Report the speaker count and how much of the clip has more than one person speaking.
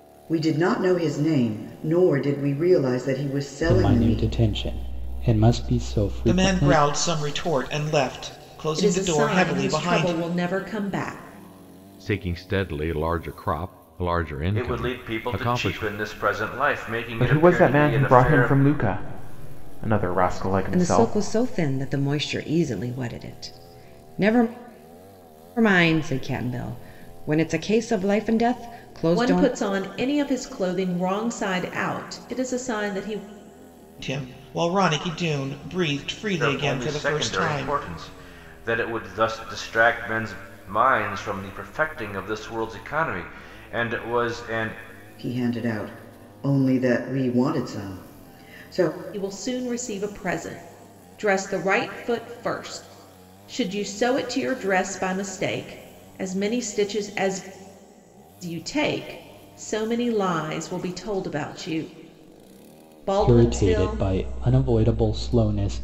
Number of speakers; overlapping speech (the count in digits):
8, about 13%